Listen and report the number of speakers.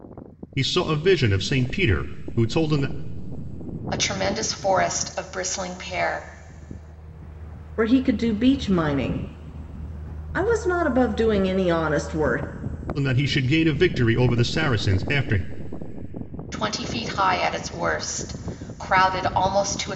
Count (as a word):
three